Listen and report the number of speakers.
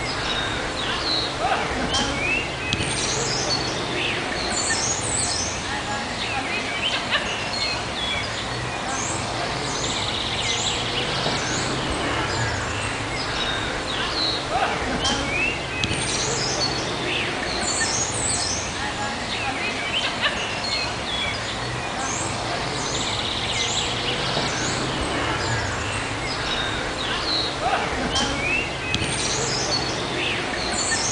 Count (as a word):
zero